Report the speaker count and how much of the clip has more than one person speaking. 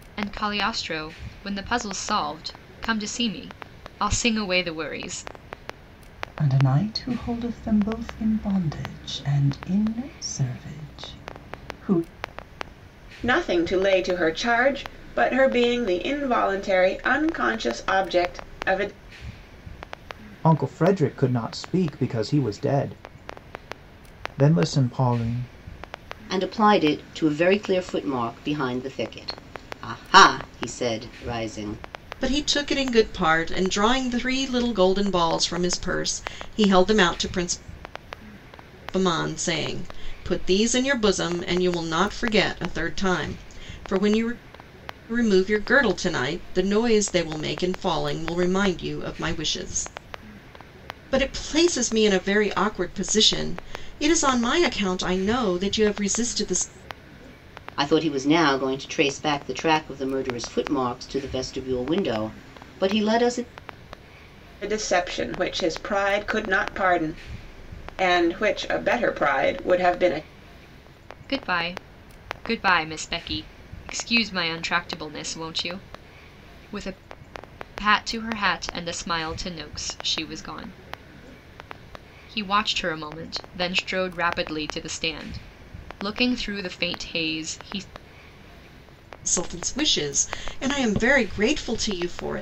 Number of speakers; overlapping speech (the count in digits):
6, no overlap